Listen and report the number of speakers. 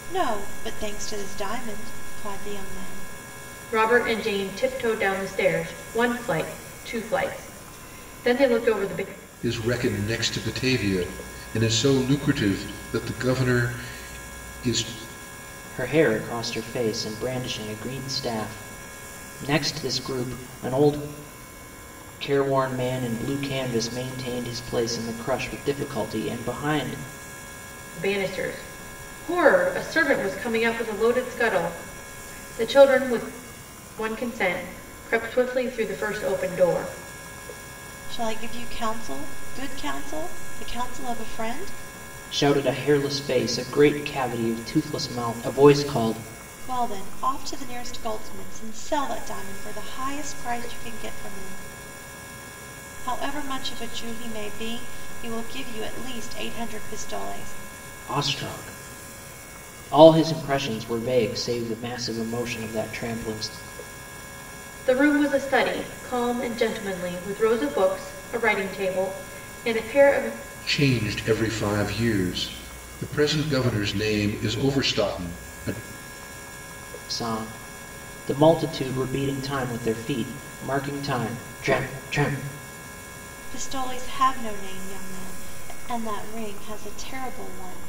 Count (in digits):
4